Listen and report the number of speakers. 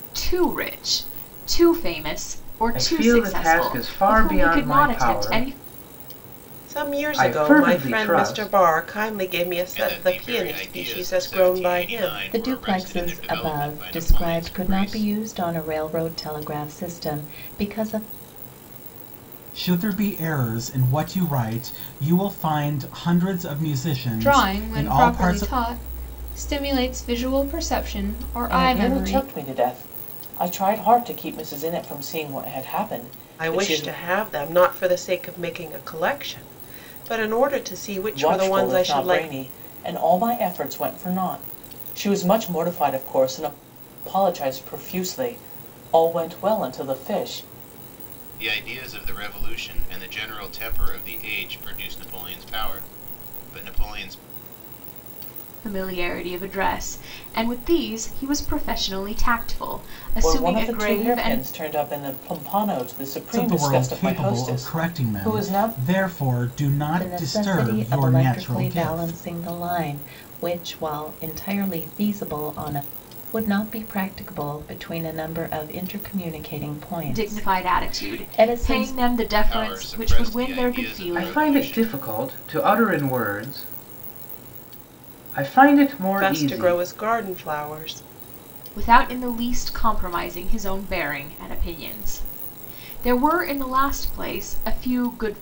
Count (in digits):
8